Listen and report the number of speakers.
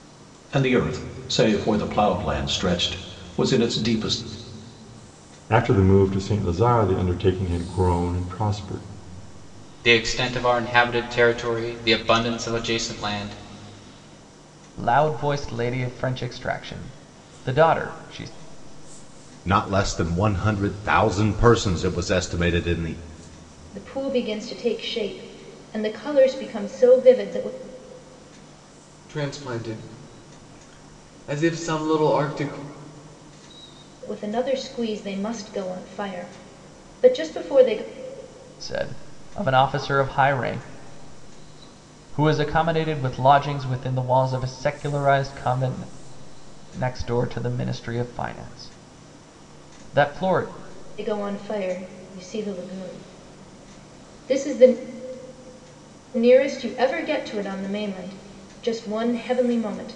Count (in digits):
7